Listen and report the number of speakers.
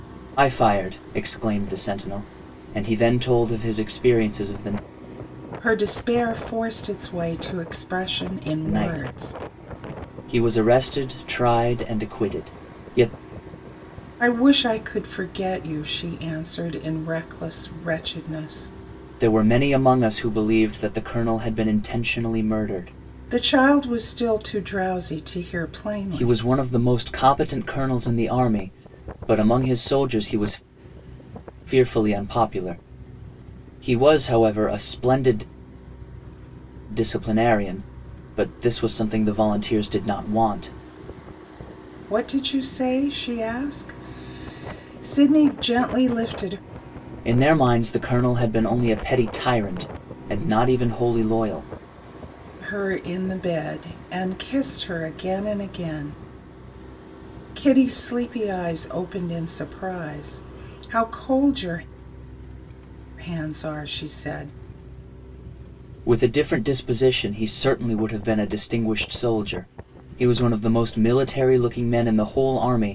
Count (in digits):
2